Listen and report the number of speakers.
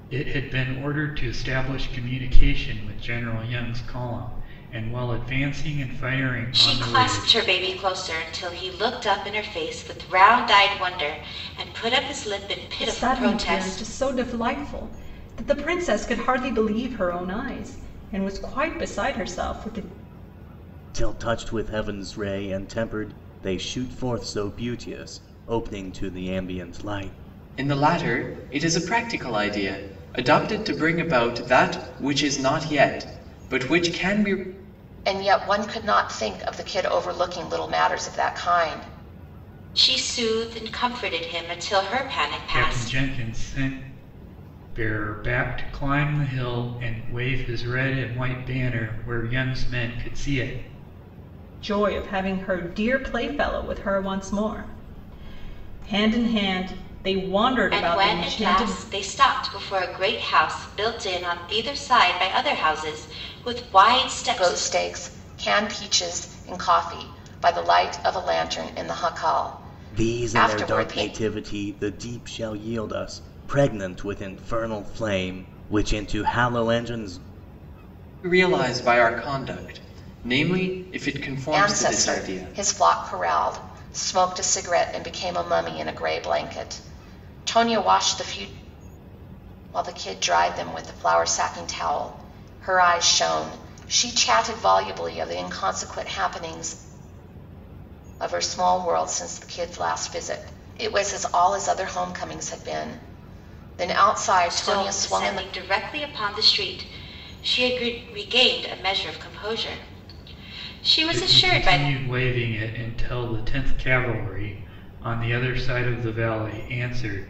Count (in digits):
6